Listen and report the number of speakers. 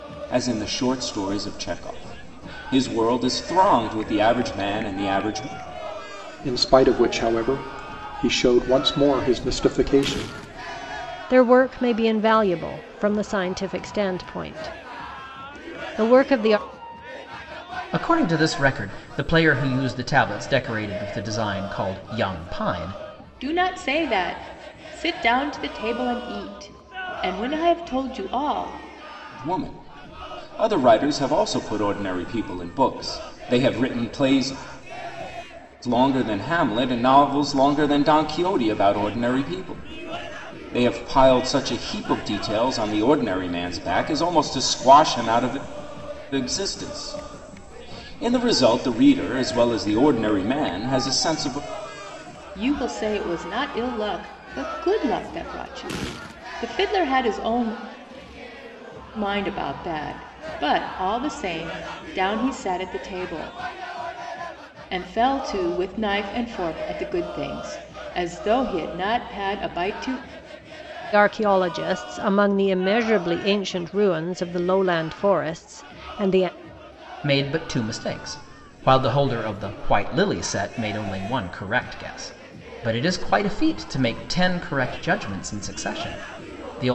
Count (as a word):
five